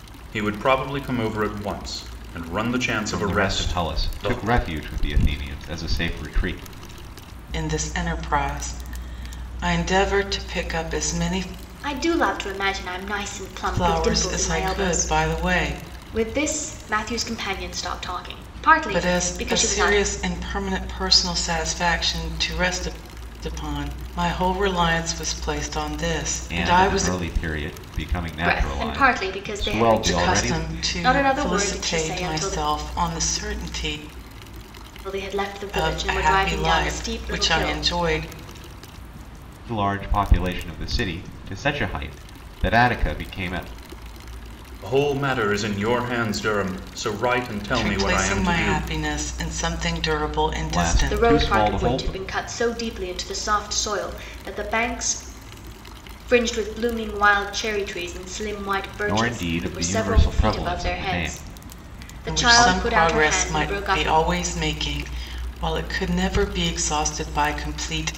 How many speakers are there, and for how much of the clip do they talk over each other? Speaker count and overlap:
4, about 28%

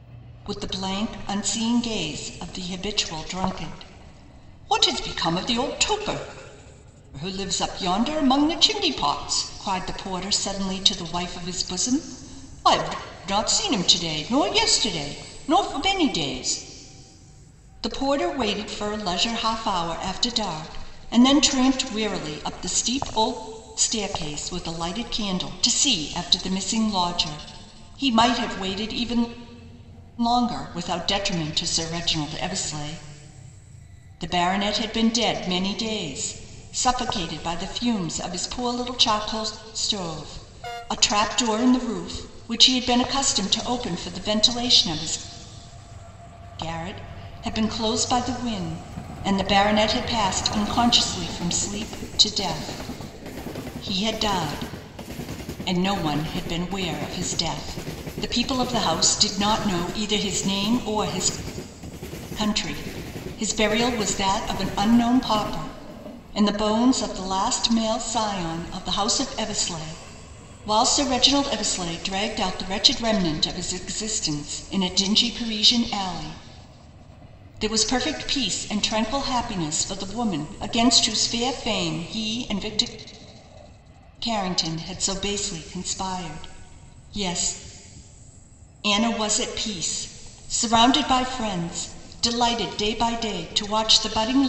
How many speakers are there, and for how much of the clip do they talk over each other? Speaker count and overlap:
1, no overlap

